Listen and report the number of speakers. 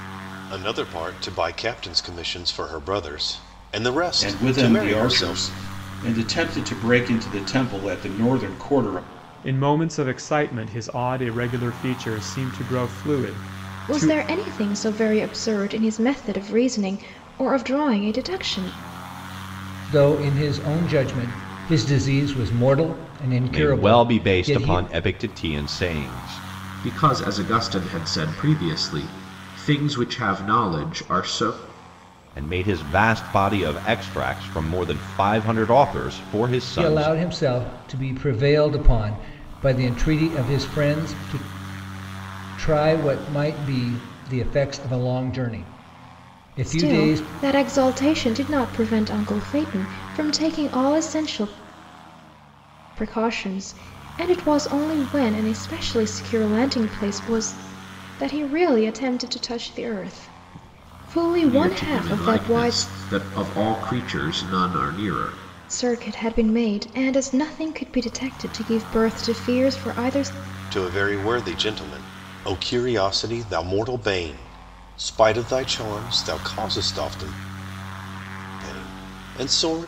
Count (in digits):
7